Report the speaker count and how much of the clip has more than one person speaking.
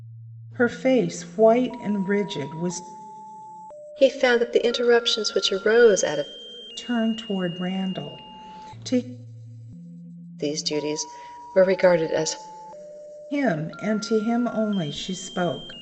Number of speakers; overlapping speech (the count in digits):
2, no overlap